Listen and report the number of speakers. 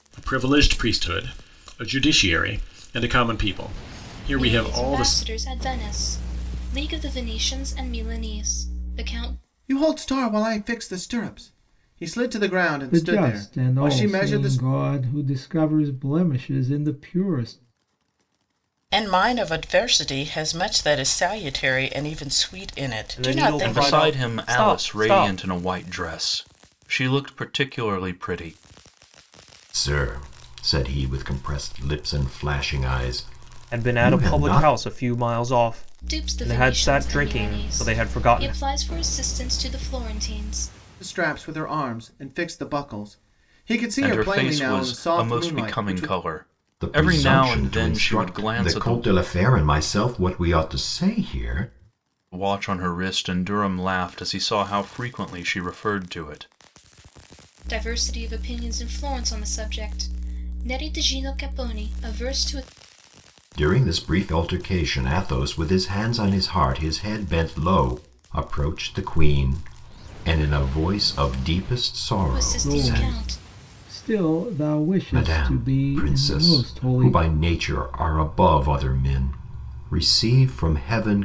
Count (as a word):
eight